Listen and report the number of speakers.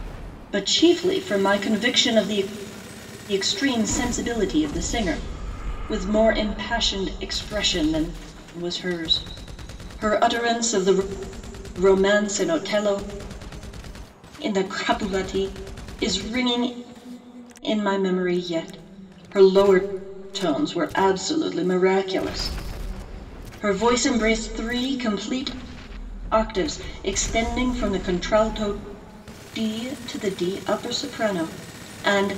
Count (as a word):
one